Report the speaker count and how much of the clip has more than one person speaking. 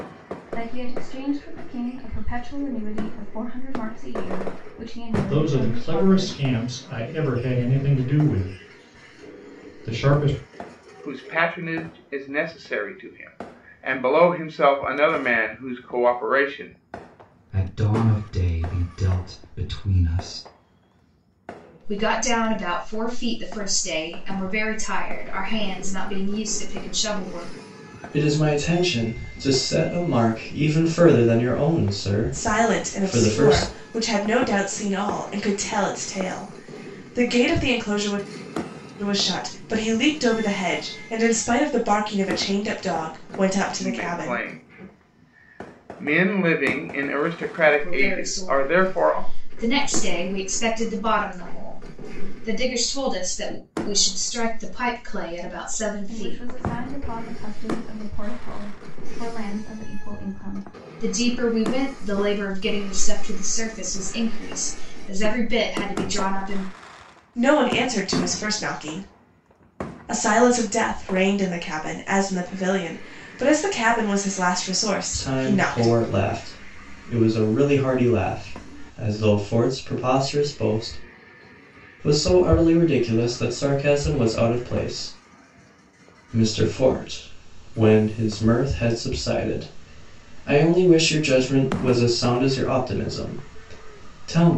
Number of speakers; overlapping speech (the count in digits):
7, about 6%